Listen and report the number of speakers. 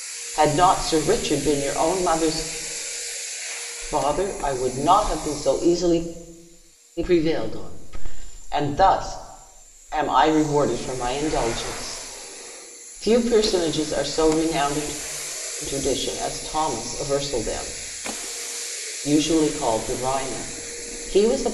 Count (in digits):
1